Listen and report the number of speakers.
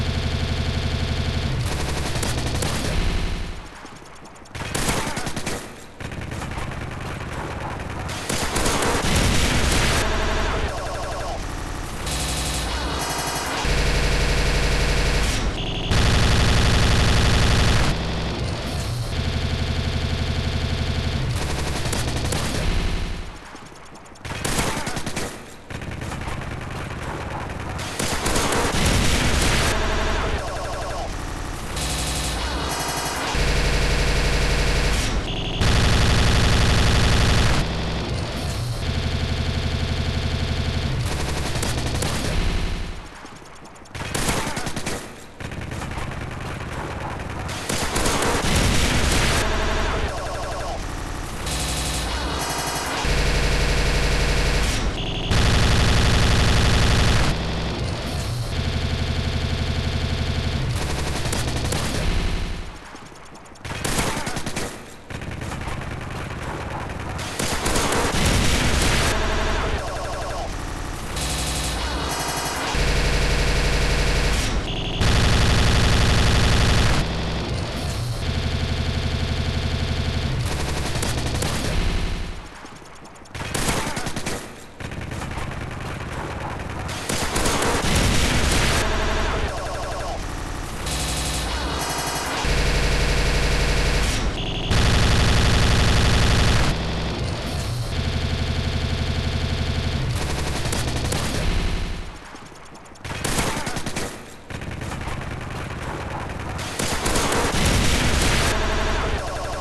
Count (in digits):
0